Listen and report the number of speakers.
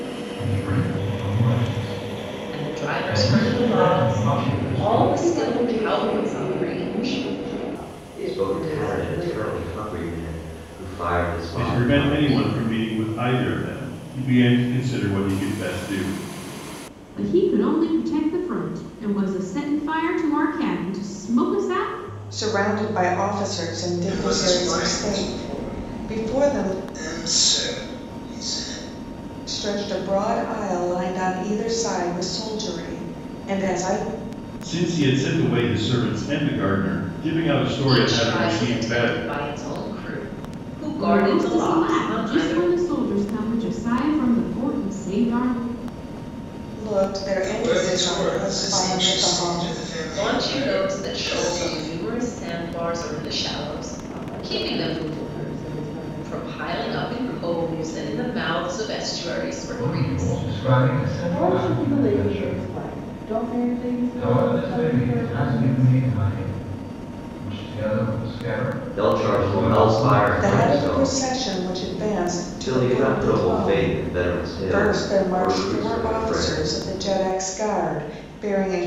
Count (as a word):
eight